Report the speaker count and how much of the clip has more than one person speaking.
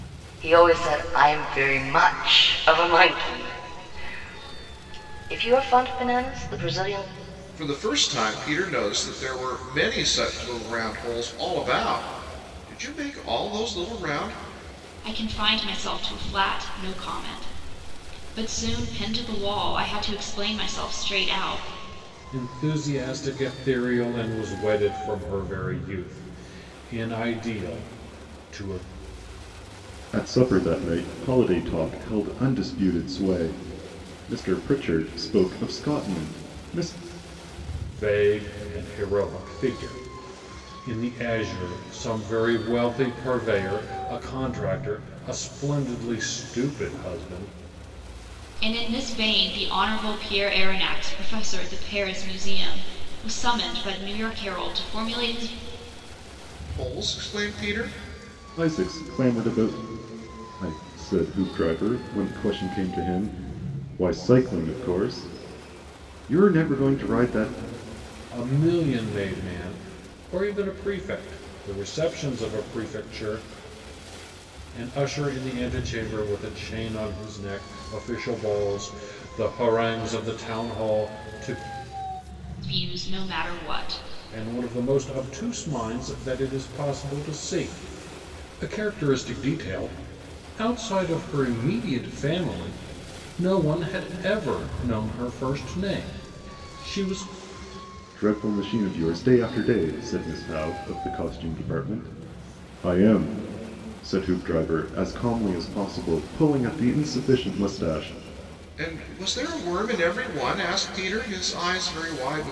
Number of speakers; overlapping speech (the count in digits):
5, no overlap